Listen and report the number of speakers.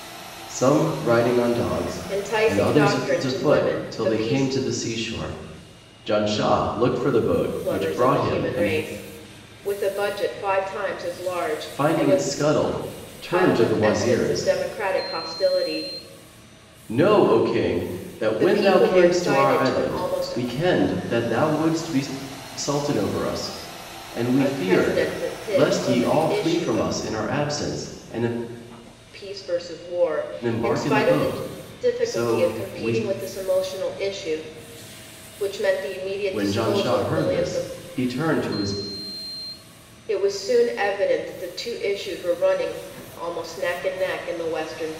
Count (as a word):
two